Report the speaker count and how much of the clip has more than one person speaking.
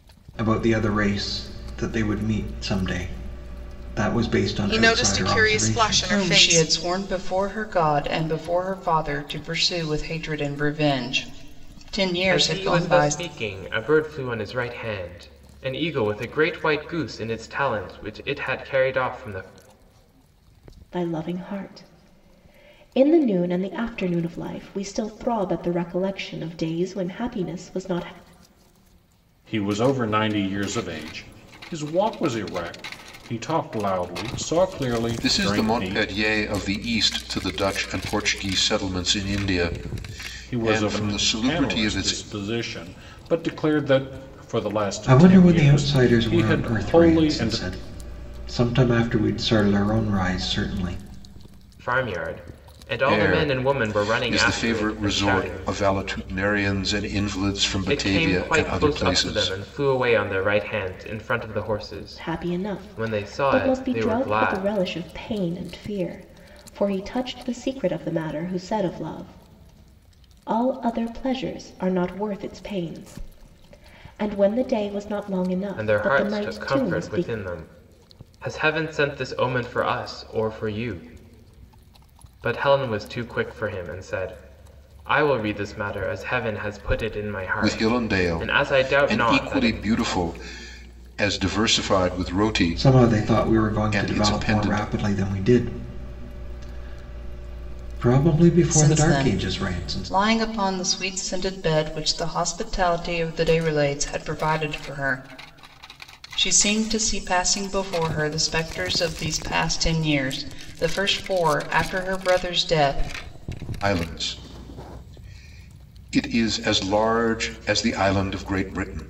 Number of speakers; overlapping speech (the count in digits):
7, about 19%